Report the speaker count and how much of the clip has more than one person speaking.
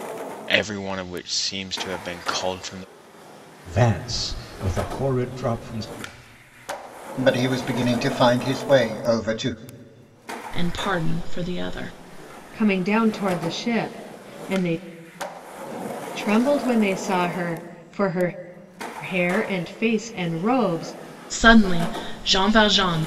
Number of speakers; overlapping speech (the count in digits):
5, no overlap